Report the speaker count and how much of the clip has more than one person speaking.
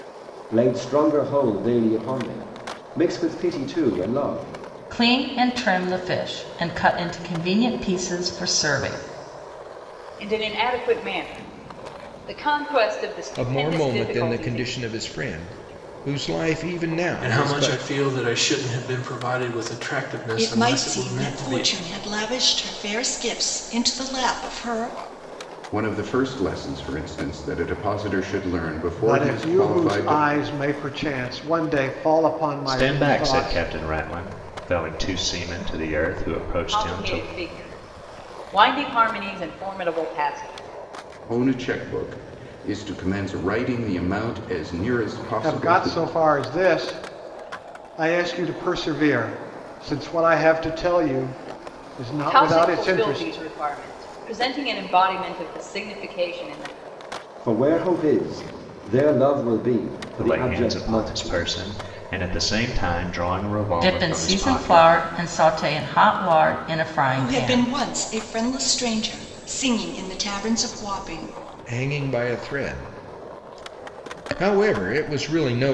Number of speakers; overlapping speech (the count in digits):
9, about 15%